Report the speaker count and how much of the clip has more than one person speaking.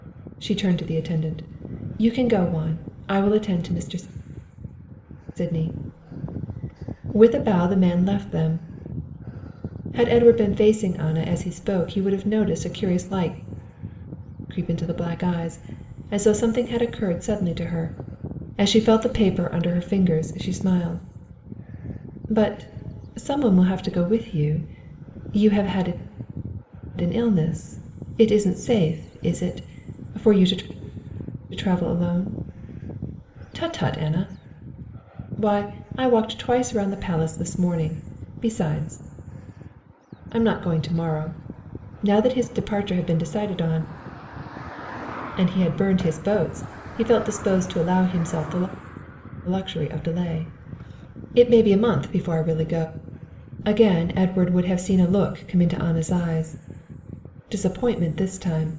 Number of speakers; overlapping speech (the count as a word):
one, no overlap